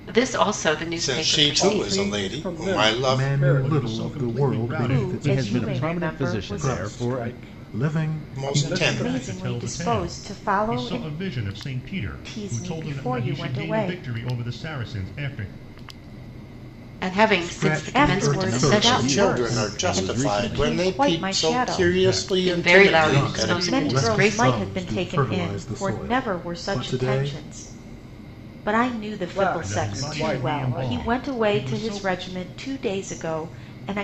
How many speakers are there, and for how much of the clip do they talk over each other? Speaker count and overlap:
7, about 71%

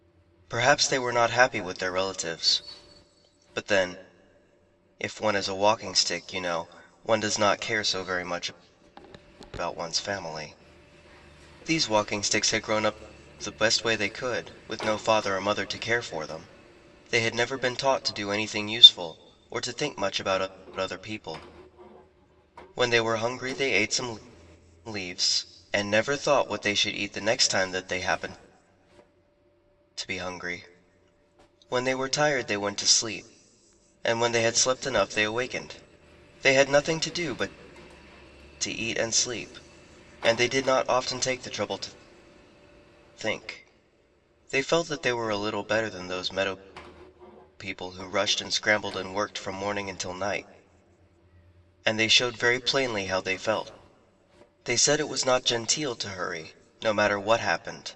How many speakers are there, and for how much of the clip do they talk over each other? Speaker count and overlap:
1, no overlap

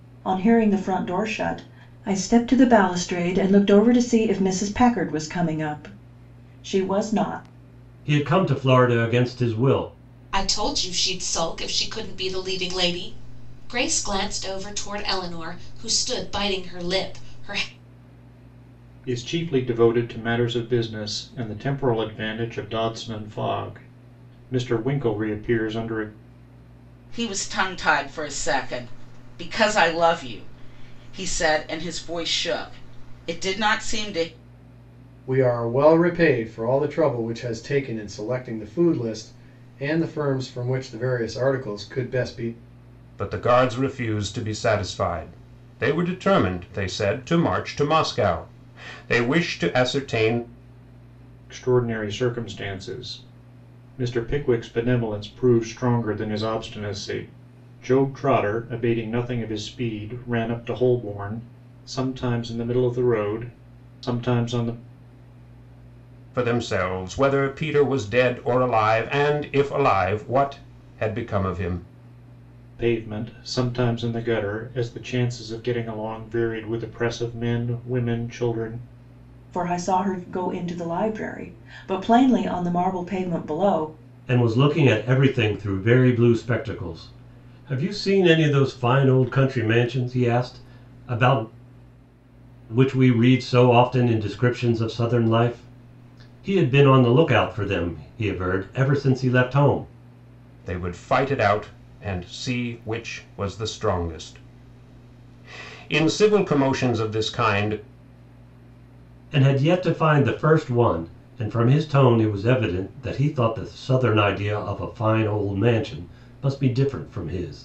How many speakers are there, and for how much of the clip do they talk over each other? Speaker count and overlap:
7, no overlap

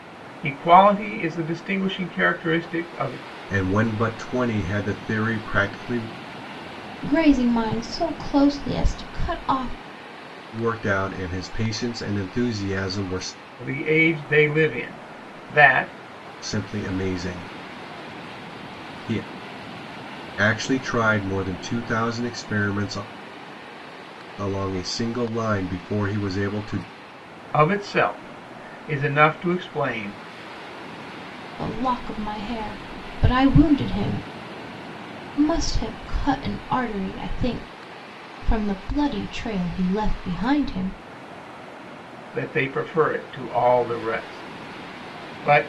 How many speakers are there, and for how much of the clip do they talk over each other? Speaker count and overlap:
3, no overlap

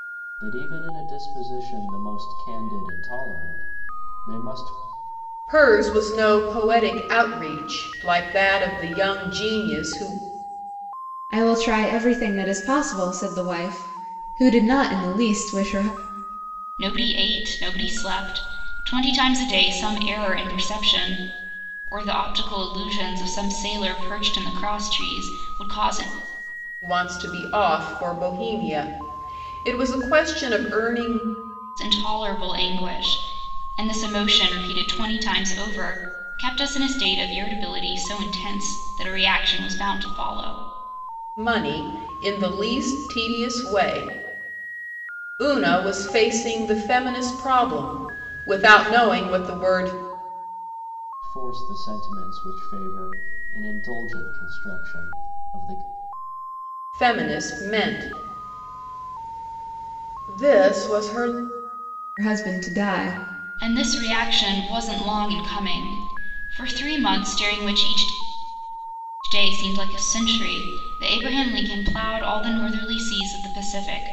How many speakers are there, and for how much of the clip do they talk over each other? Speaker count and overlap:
4, no overlap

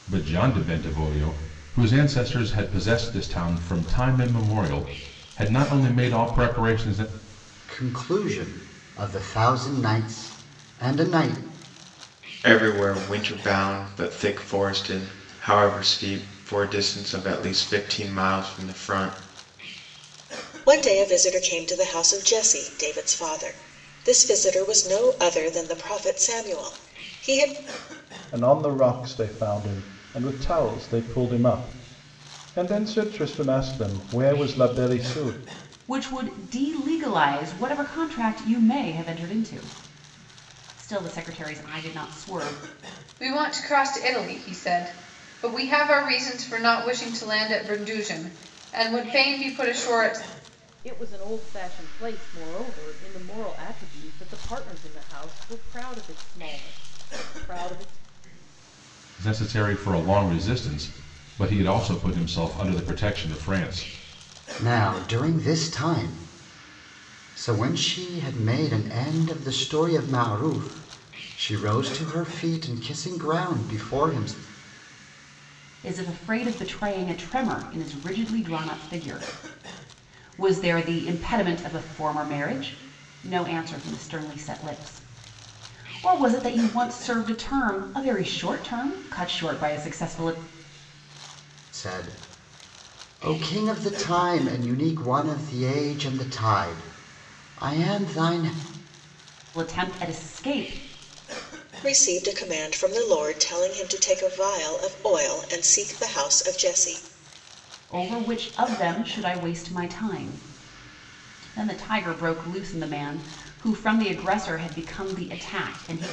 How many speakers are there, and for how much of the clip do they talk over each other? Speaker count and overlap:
8, no overlap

